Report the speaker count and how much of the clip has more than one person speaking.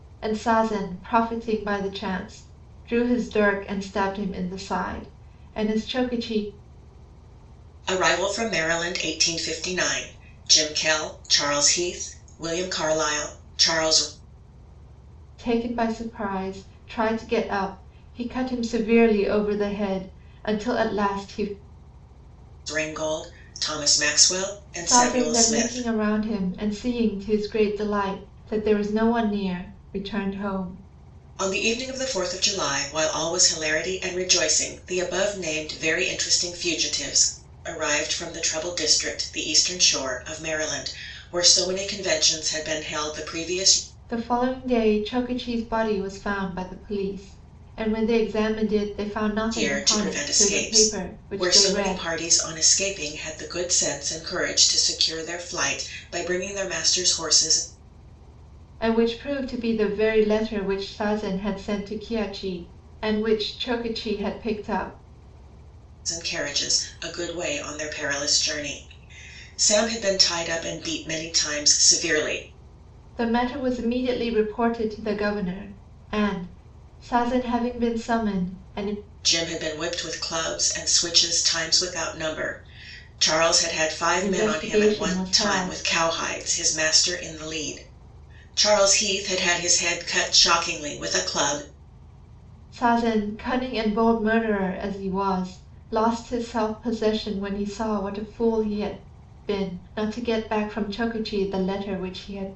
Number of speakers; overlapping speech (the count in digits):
2, about 5%